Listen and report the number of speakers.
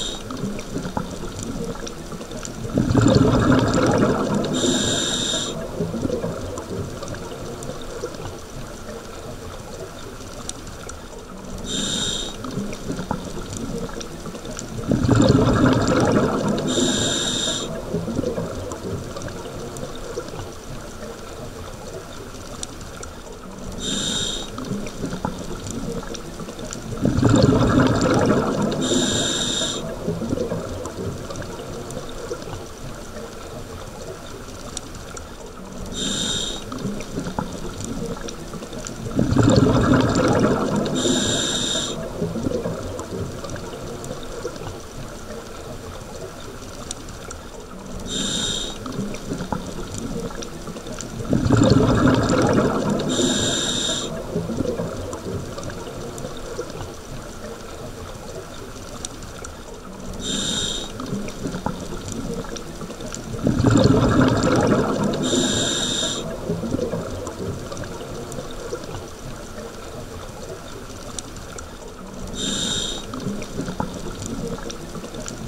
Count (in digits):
0